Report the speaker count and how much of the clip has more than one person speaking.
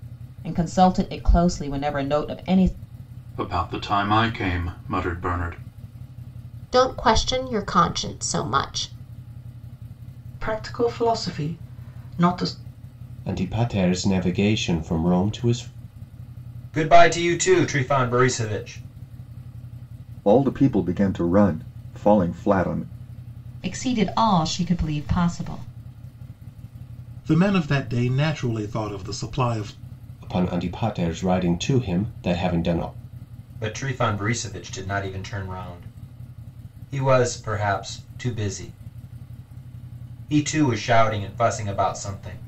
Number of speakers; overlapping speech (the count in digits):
9, no overlap